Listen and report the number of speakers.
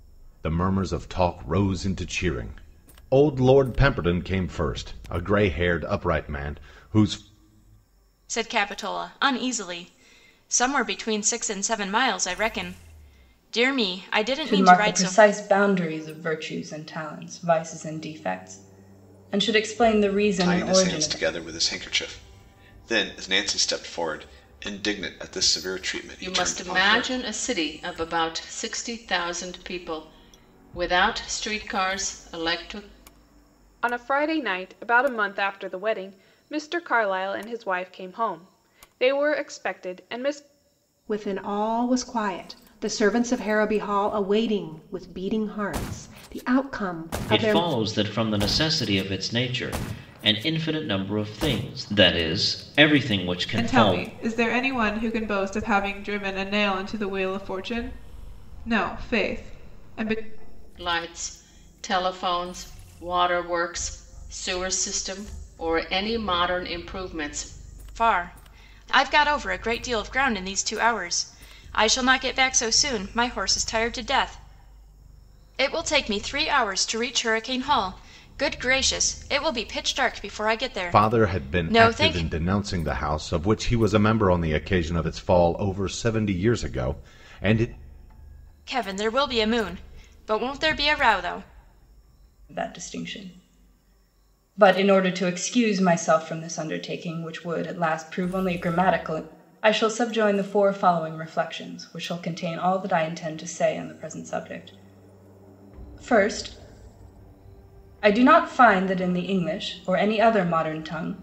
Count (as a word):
nine